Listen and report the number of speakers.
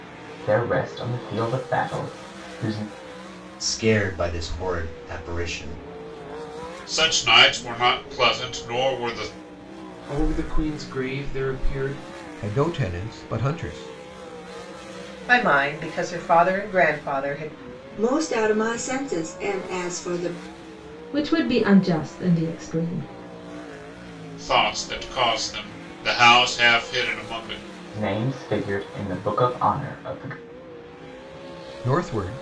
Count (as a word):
eight